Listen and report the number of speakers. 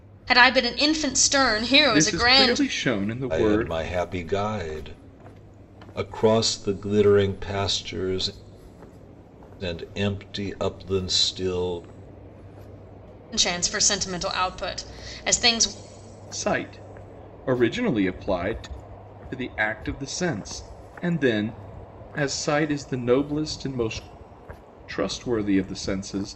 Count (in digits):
3